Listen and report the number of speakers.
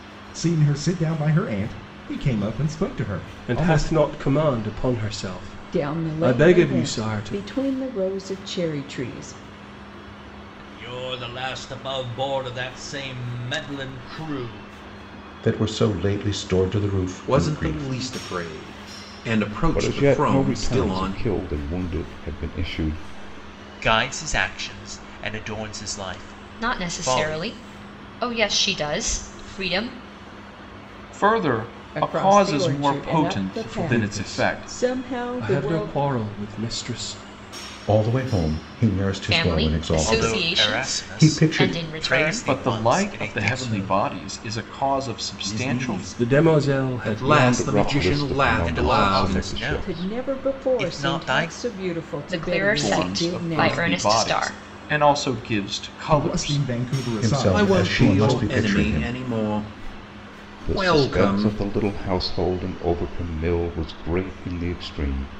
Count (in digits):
10